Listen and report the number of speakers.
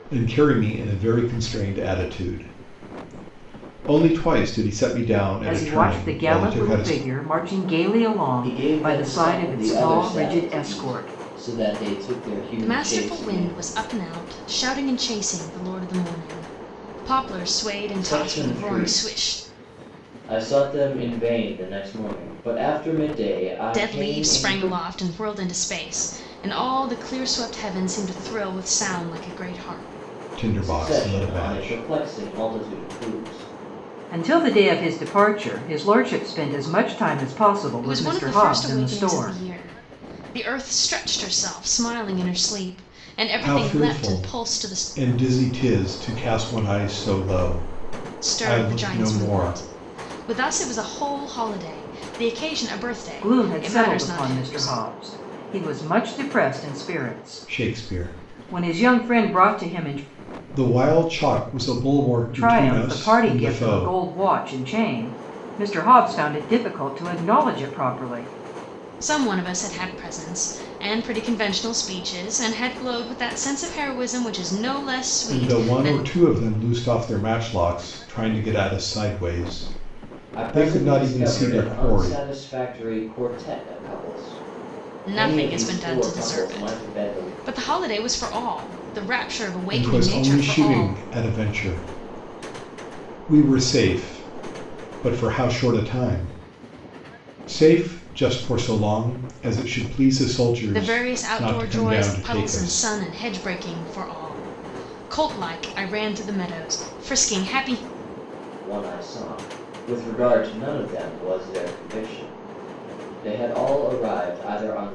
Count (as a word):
four